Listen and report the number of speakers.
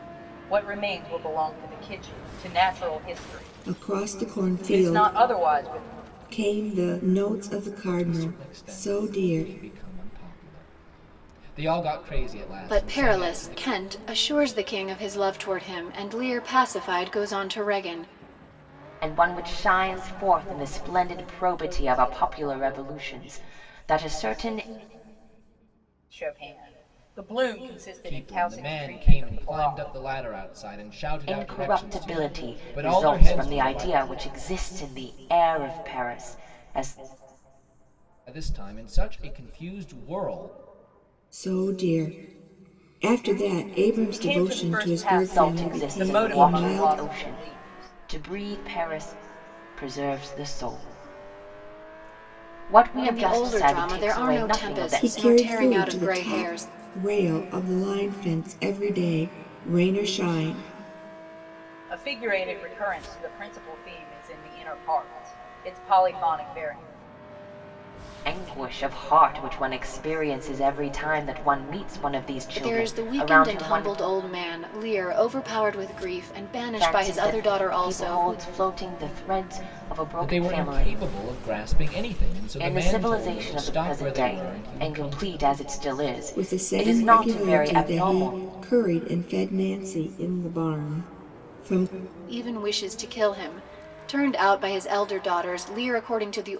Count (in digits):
5